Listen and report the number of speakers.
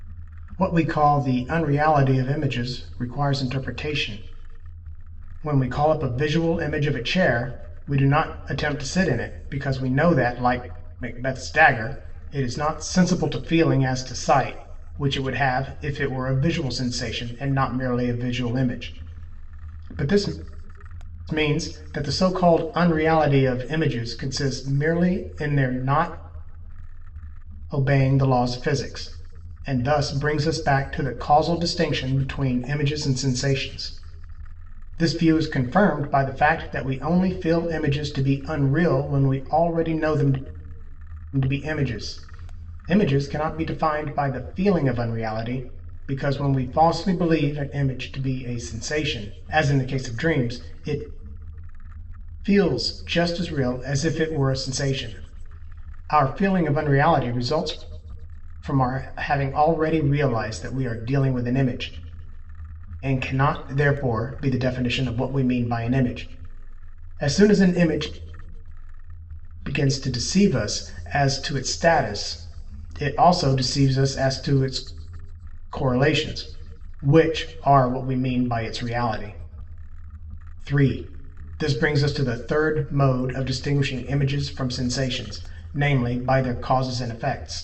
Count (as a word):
one